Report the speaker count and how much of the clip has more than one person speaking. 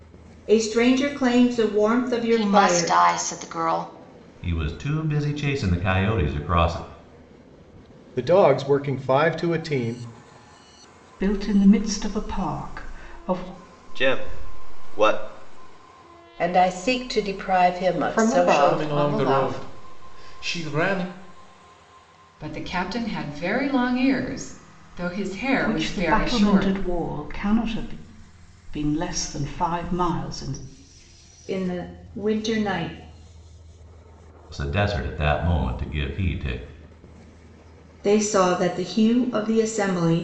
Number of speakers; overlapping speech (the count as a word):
ten, about 9%